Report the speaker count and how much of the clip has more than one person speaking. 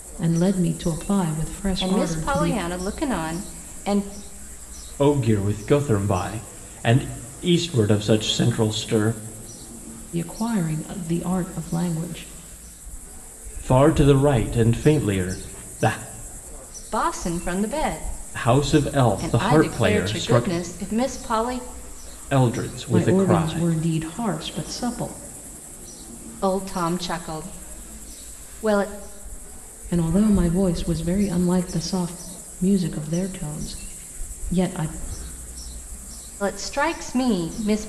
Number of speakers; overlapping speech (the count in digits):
3, about 8%